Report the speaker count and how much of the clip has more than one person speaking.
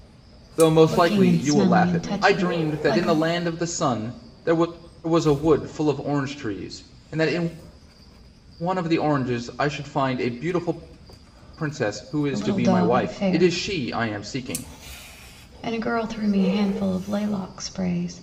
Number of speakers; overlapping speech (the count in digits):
2, about 19%